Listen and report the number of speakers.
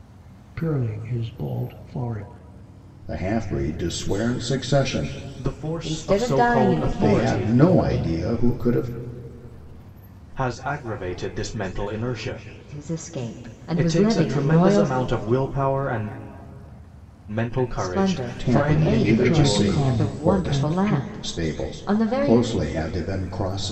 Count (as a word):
four